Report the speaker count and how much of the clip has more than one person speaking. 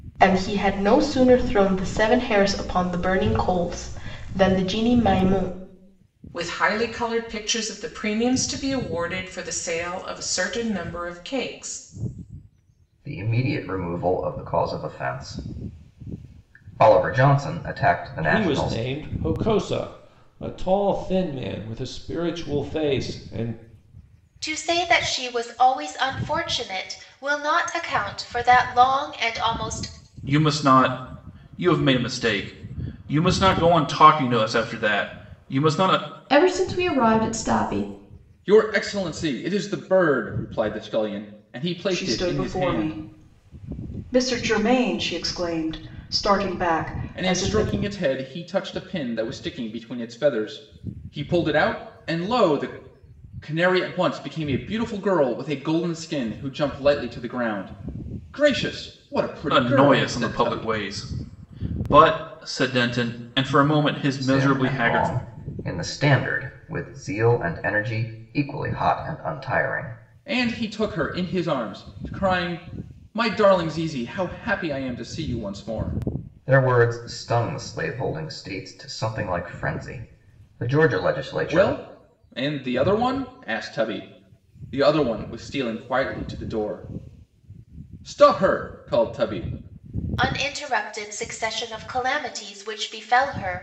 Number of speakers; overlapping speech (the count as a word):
nine, about 5%